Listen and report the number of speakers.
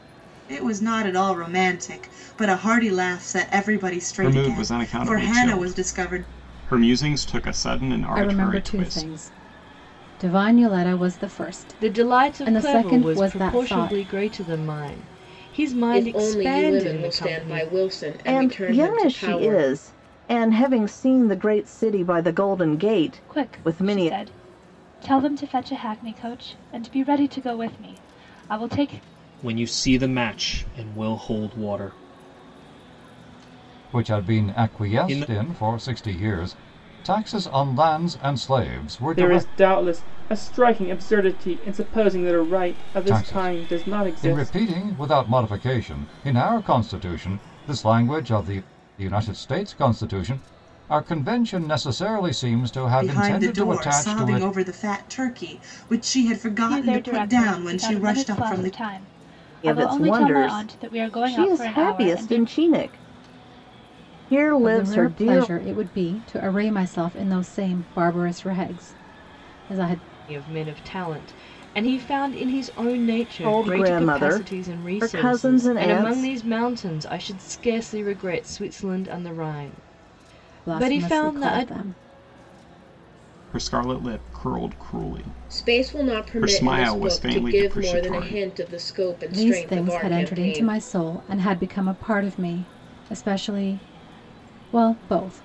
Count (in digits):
10